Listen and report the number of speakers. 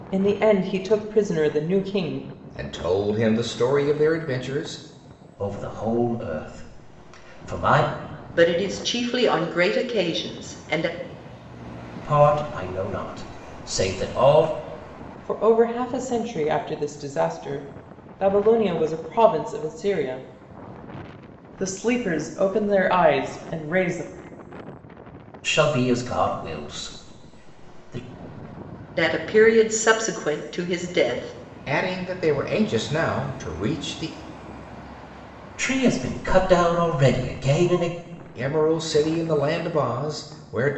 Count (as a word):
four